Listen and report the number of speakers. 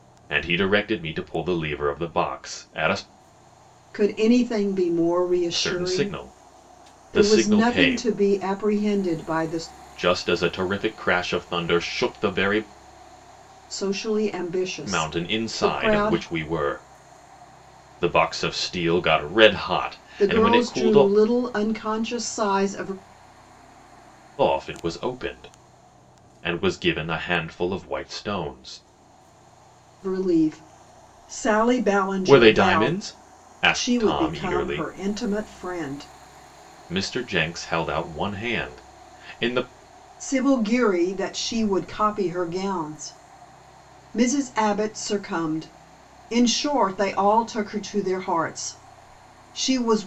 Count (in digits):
2